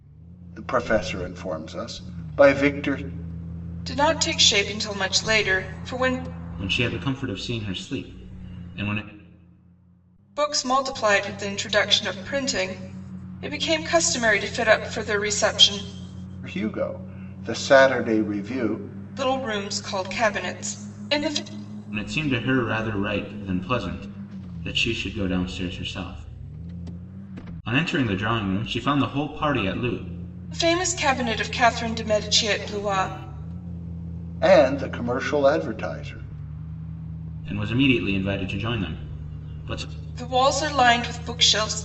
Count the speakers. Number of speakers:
3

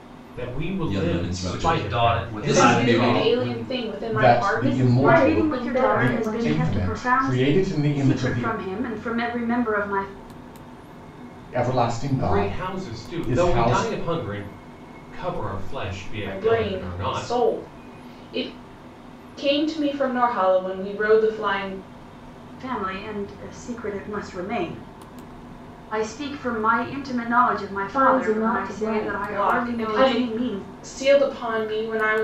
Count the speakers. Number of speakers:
7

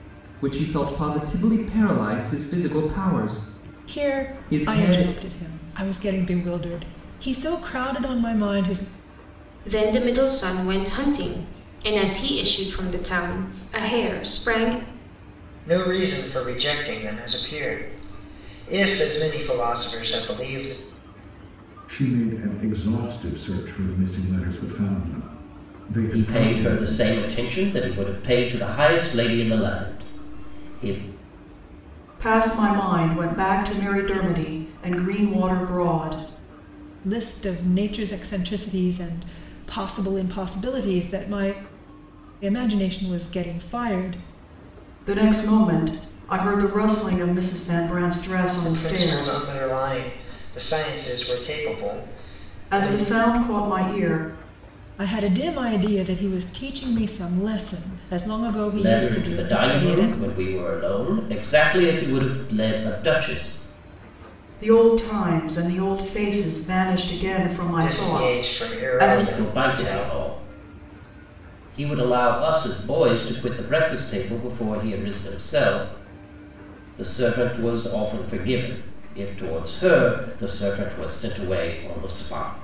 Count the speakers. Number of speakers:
7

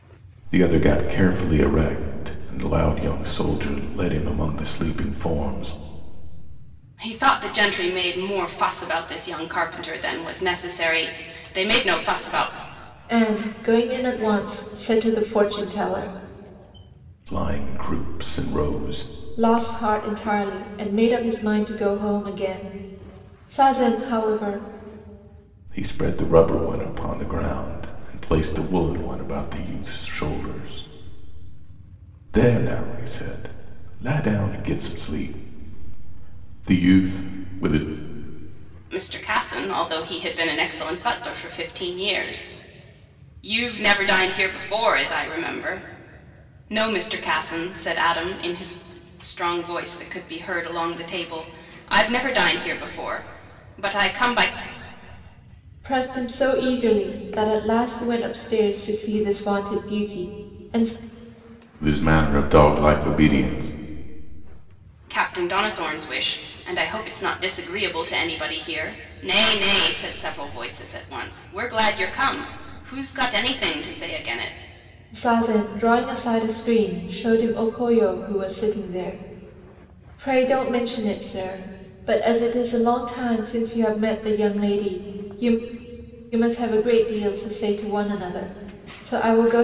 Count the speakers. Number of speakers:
3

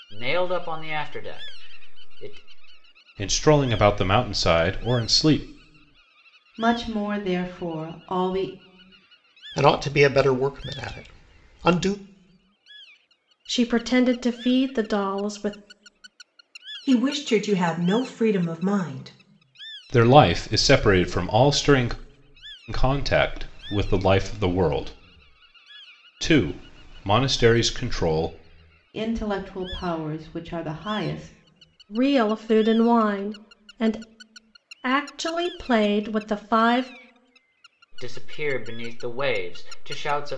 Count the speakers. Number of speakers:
6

